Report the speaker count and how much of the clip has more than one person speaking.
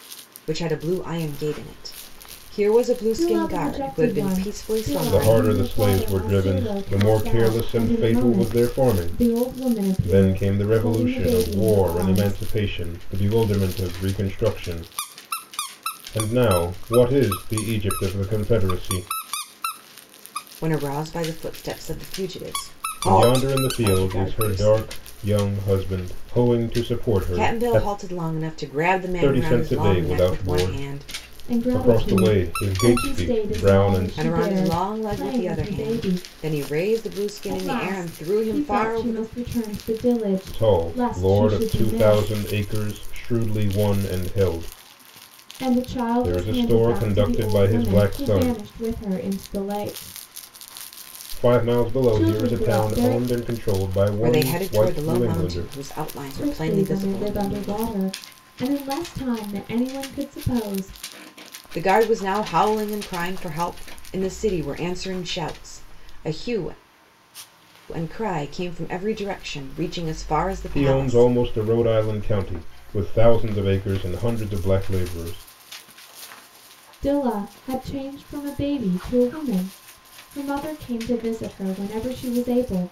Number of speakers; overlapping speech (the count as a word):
three, about 36%